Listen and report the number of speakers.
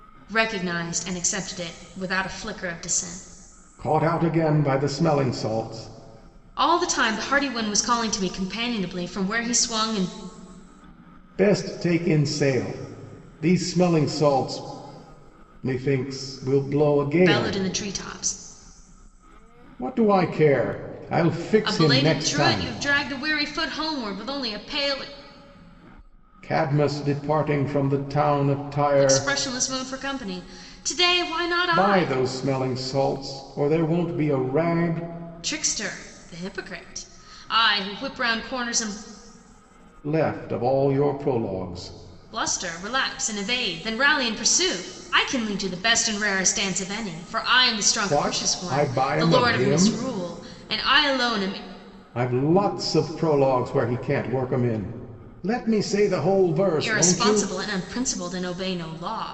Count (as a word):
two